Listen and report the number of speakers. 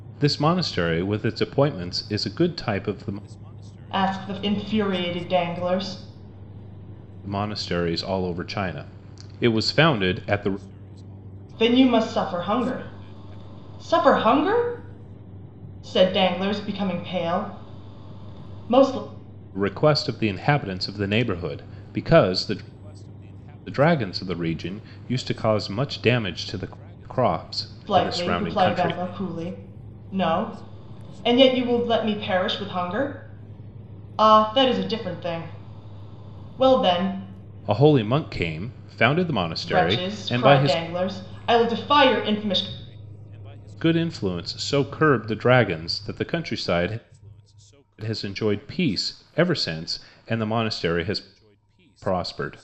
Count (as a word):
two